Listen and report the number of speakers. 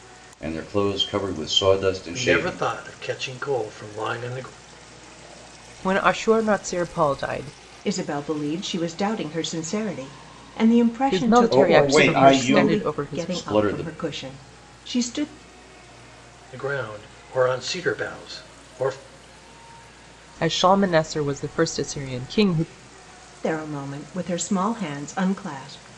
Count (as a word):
four